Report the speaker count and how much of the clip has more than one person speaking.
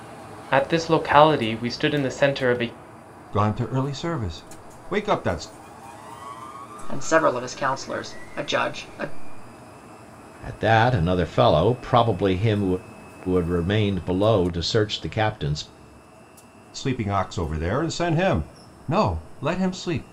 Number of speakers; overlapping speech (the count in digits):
4, no overlap